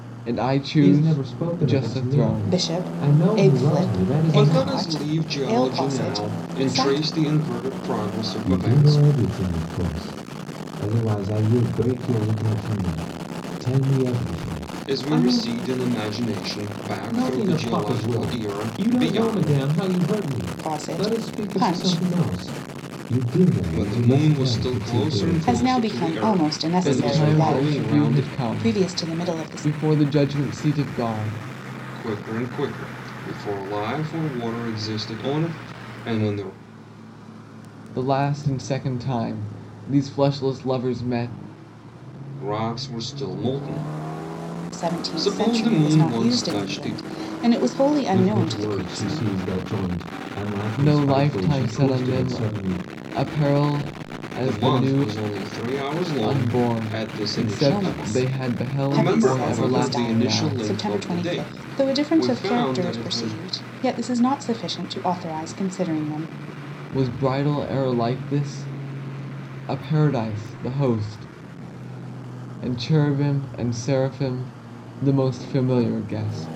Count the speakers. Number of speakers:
four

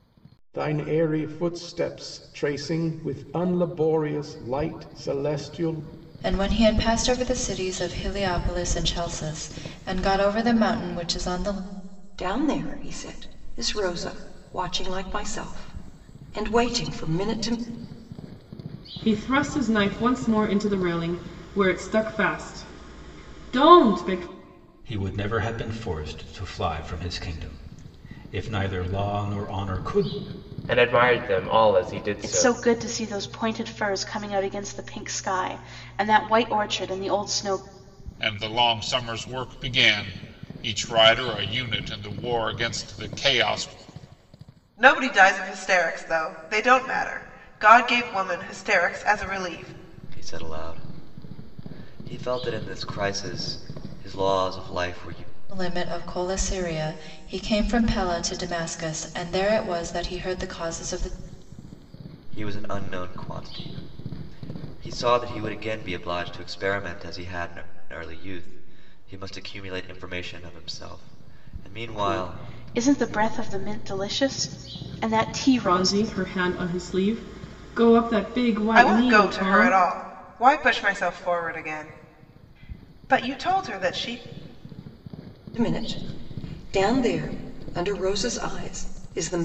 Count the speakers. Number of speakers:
ten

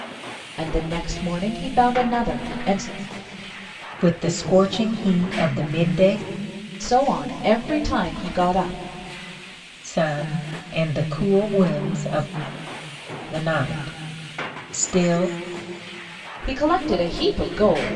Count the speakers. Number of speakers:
two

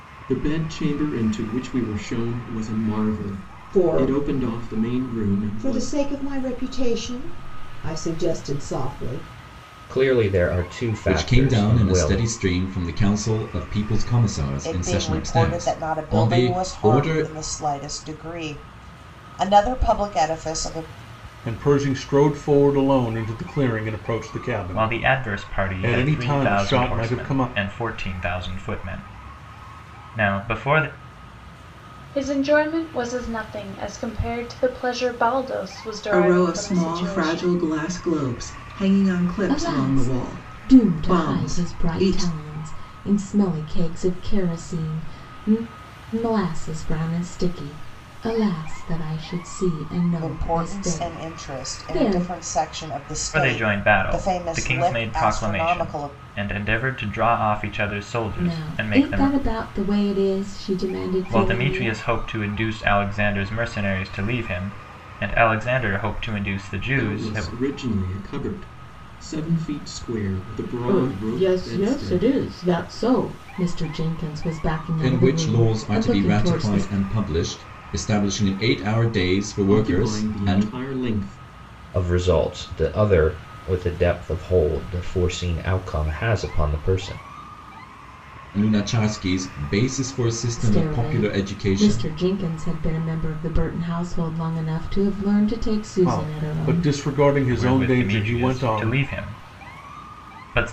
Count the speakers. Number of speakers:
ten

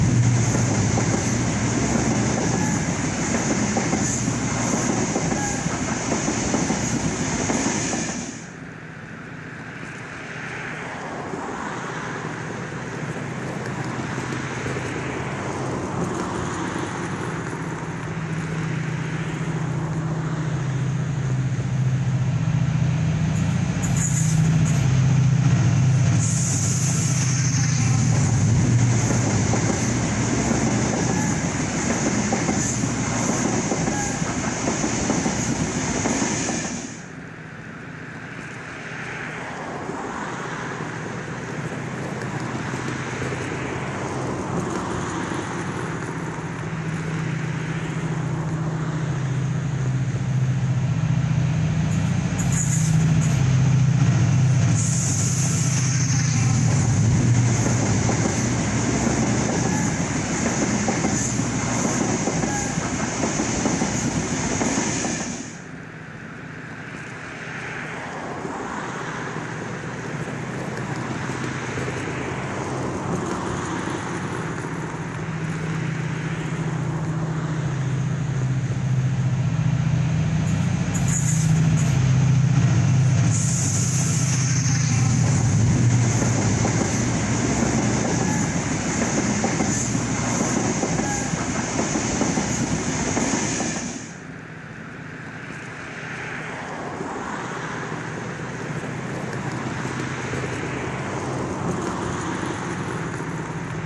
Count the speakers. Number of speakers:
zero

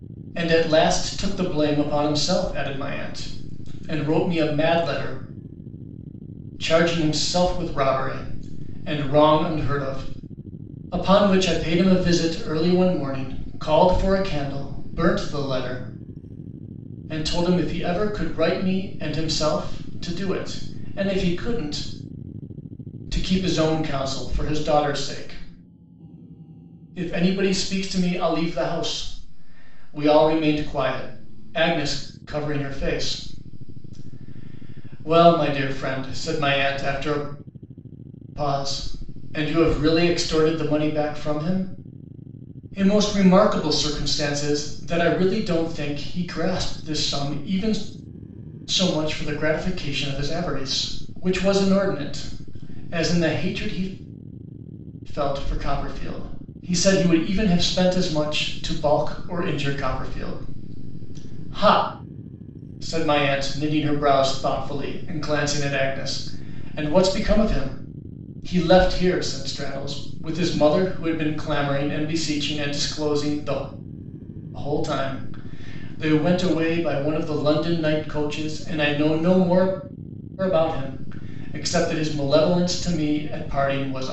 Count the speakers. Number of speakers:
one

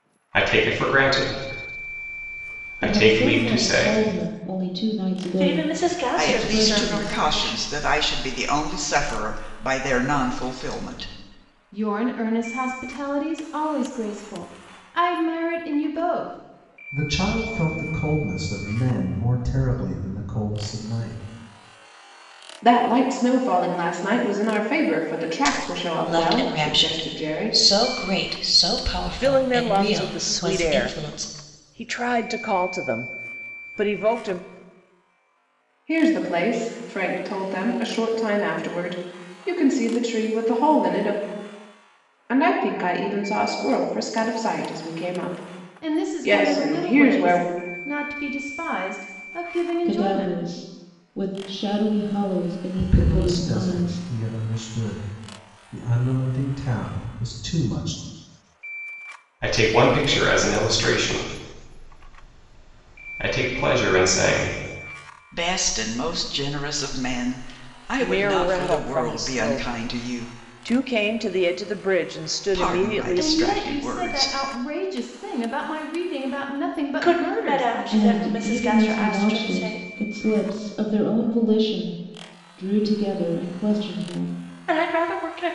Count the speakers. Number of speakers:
nine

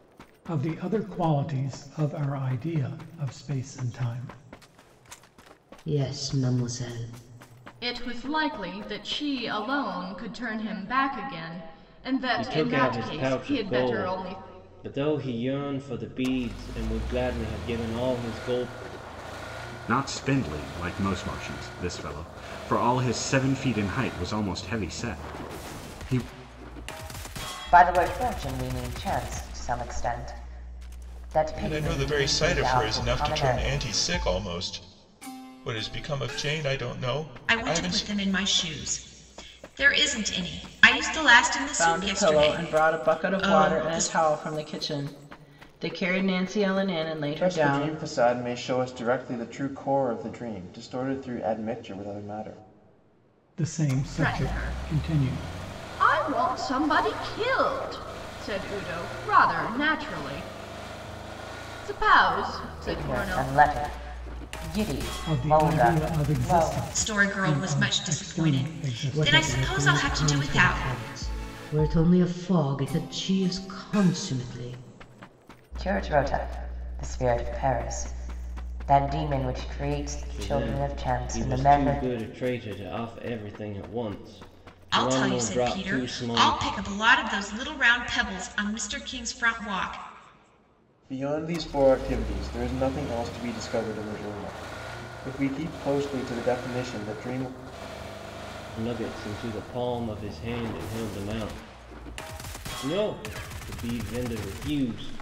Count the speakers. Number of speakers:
ten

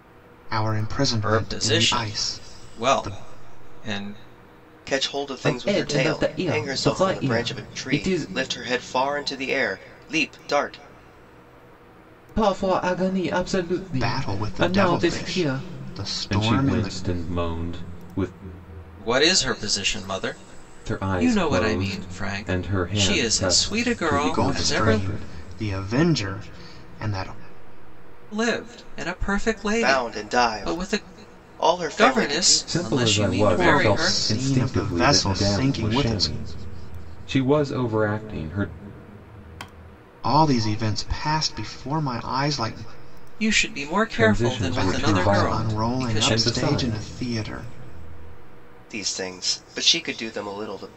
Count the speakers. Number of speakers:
four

